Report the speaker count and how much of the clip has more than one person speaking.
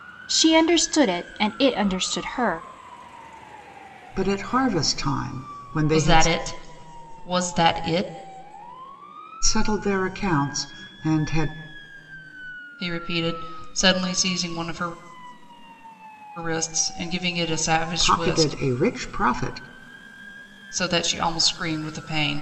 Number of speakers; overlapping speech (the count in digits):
3, about 5%